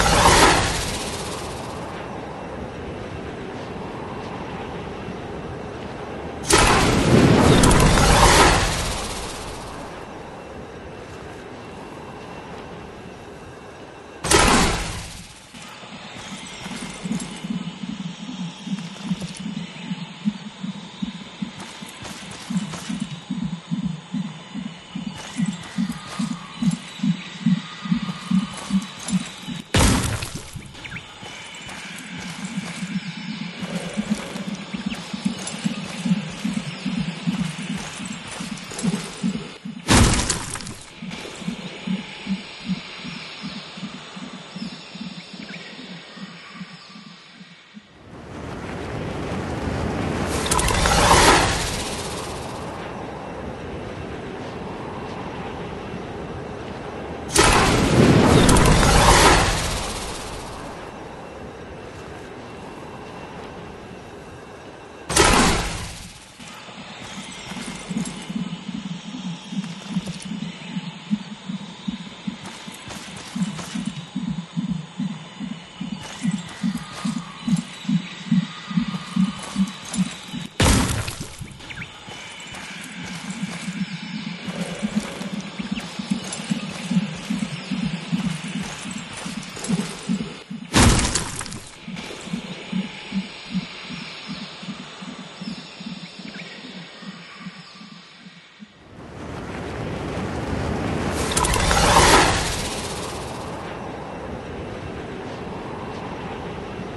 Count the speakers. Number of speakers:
0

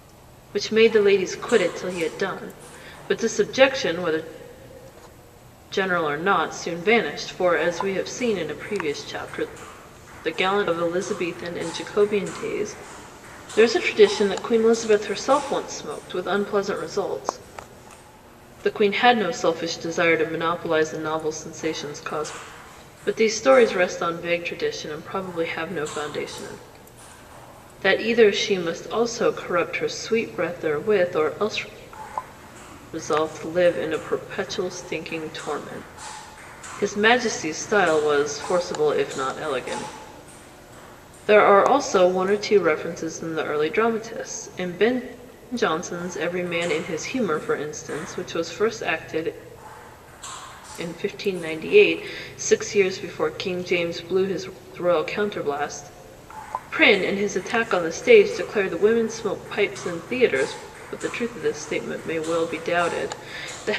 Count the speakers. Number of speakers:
1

